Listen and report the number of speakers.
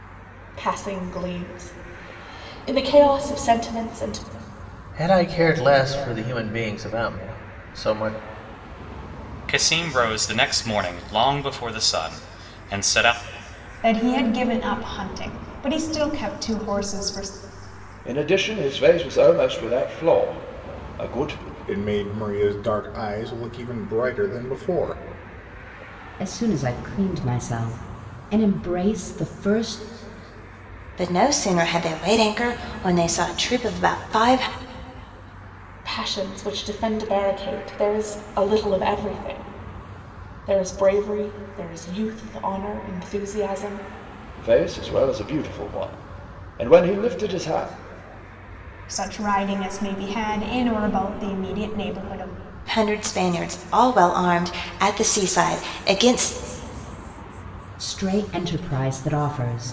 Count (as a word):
eight